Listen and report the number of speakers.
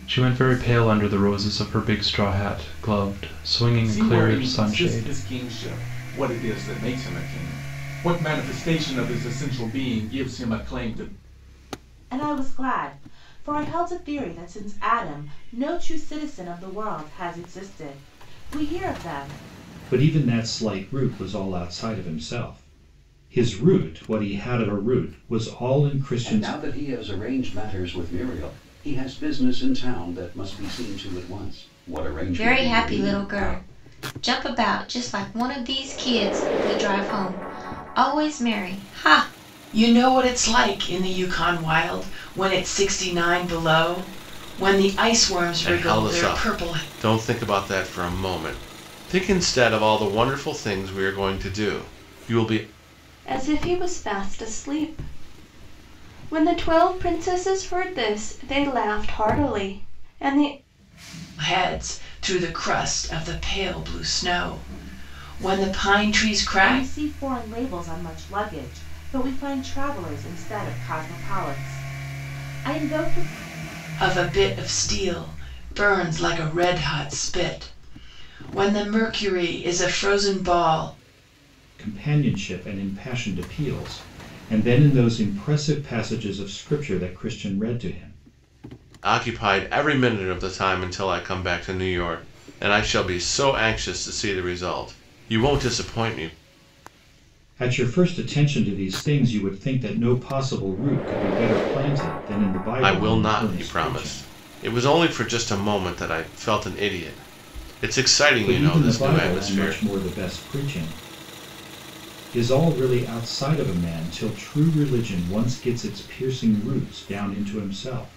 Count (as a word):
nine